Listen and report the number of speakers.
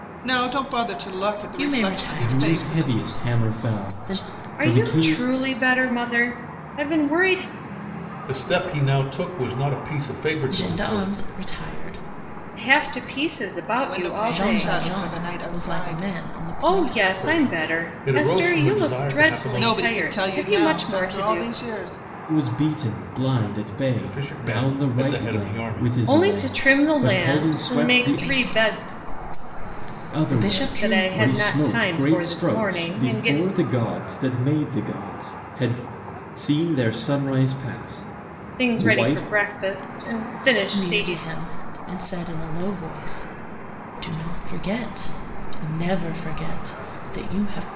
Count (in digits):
5